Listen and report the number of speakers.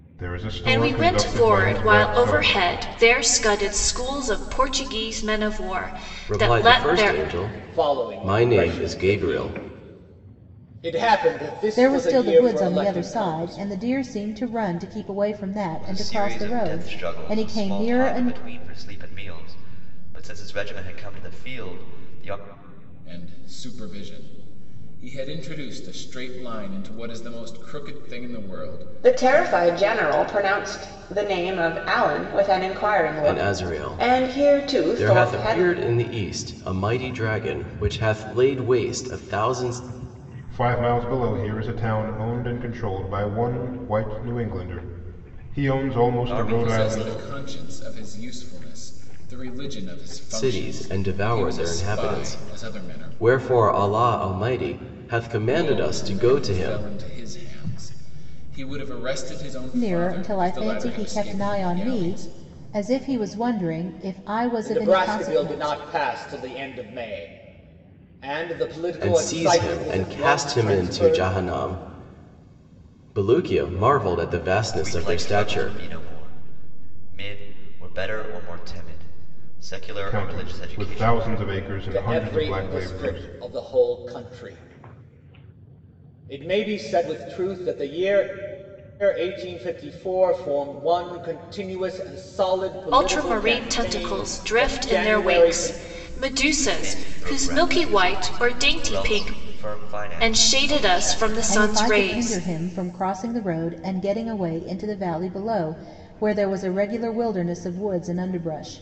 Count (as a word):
eight